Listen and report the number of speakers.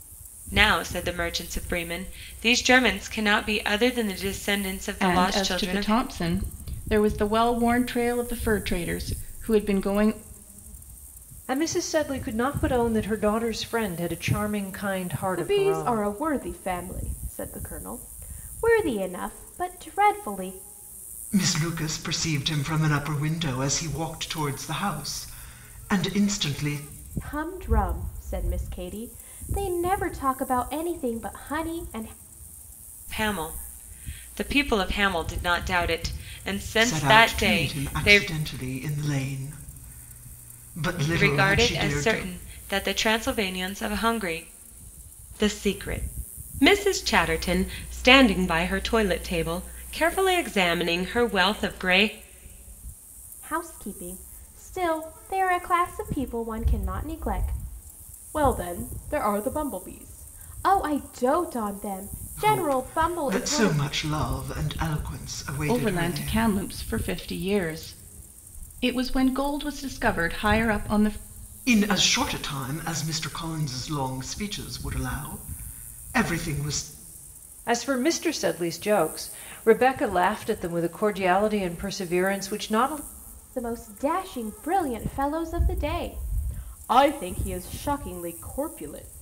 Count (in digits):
5